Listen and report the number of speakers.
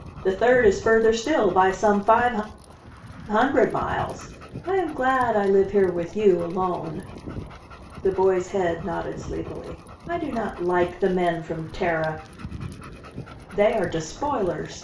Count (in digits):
1